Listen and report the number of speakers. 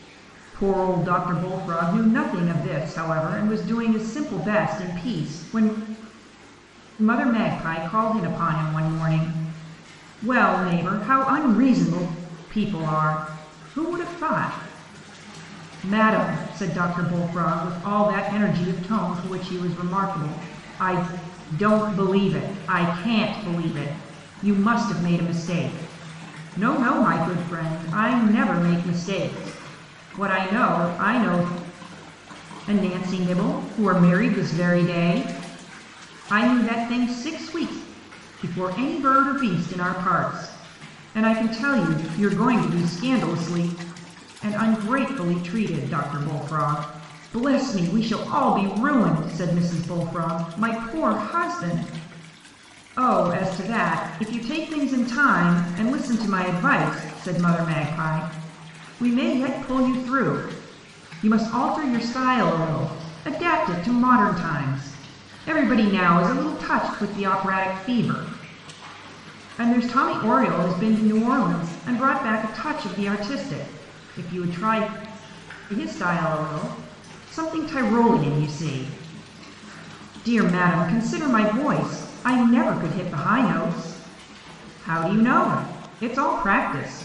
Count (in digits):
1